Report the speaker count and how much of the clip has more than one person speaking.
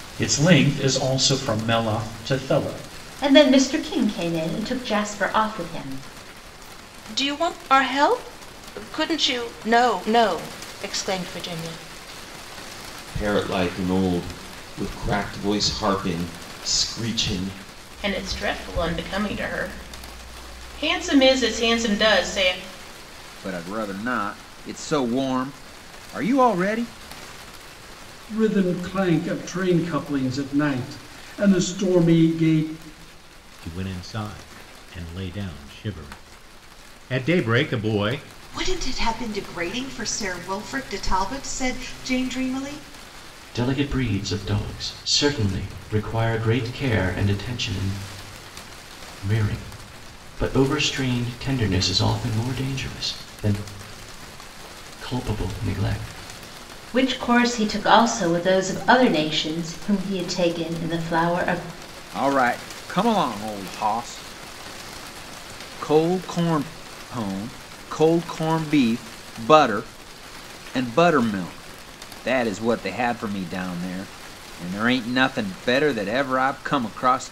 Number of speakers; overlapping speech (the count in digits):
10, no overlap